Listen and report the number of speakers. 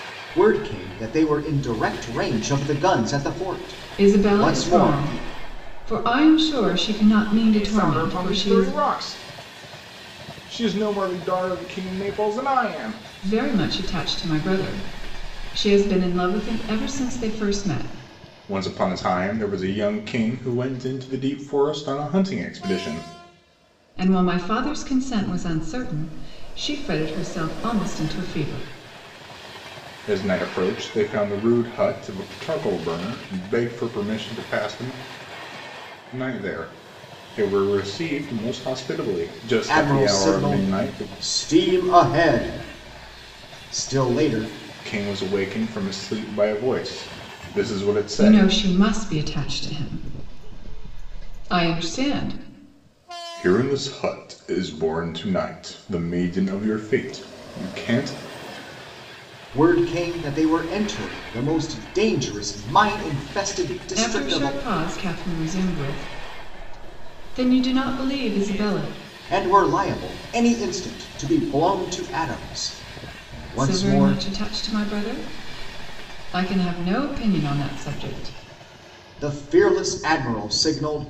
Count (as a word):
three